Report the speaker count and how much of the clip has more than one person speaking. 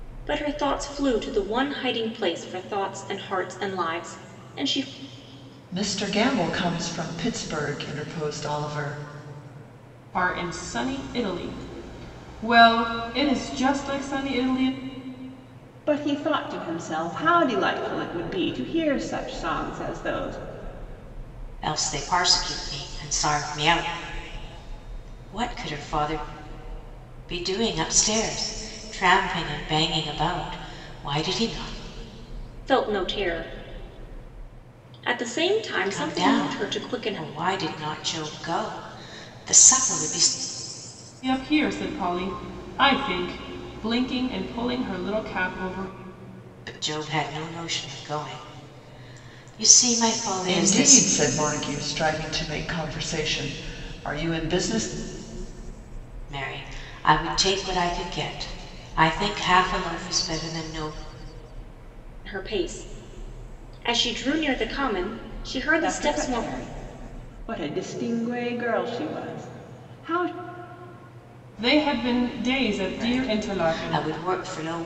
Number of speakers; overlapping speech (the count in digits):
5, about 5%